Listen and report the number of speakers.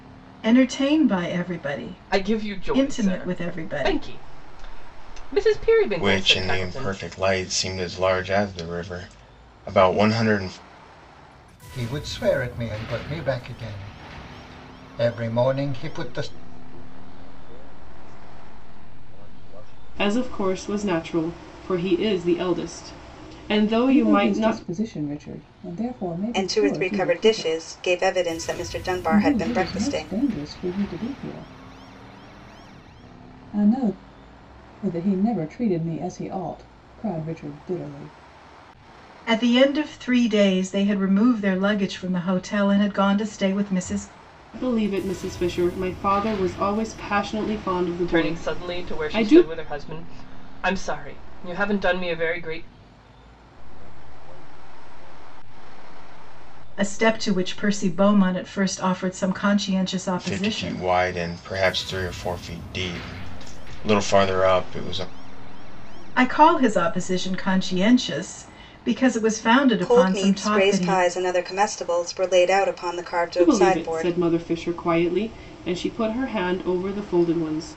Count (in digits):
8